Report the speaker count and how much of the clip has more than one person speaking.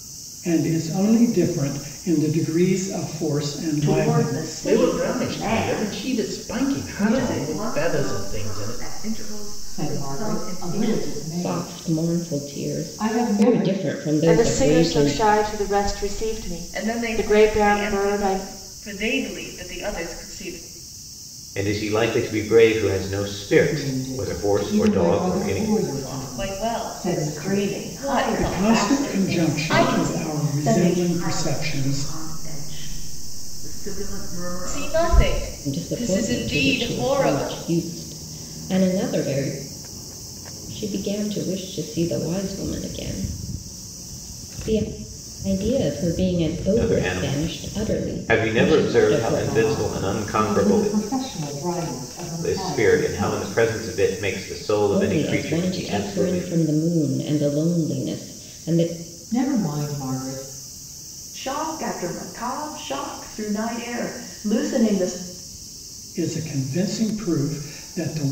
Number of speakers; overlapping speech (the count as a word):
nine, about 43%